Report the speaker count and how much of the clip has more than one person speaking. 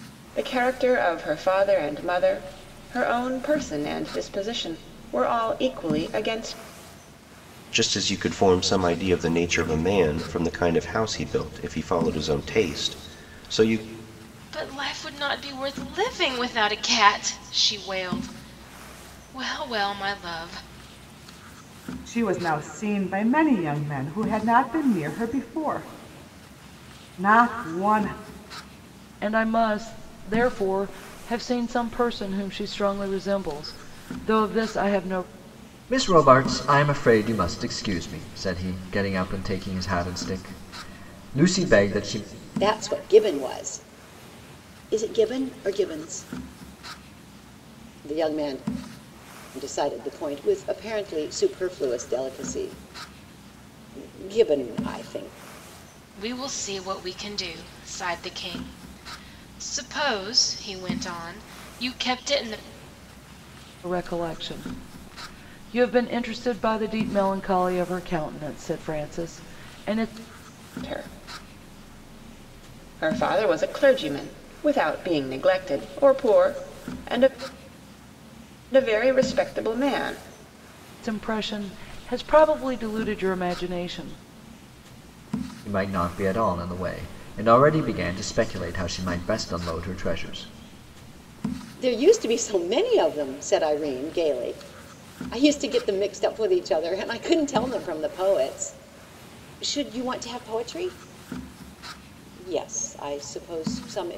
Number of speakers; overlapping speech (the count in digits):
7, no overlap